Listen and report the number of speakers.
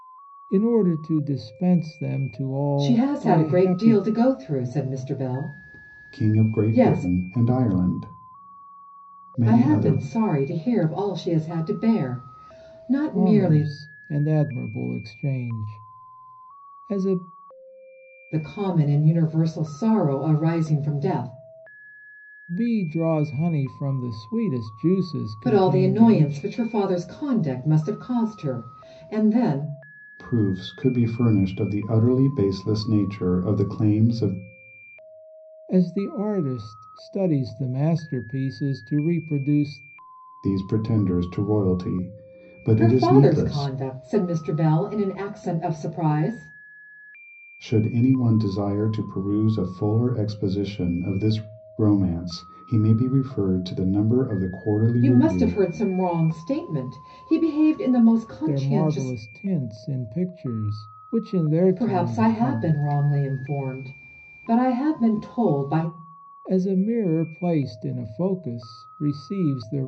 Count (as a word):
three